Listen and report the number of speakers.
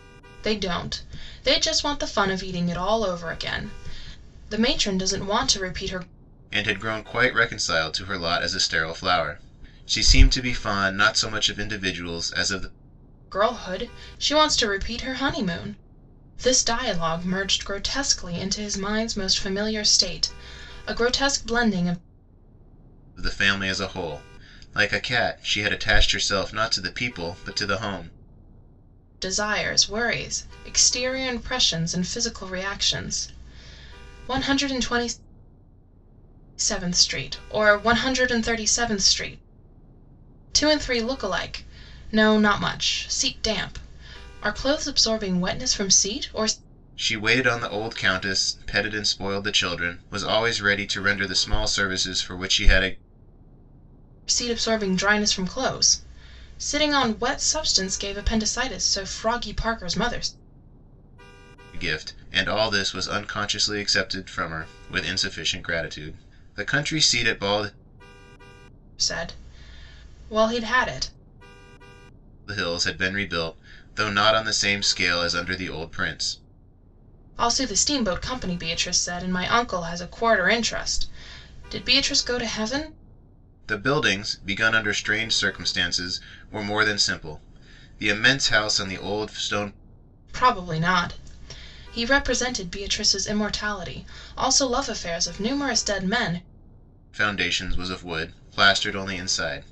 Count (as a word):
two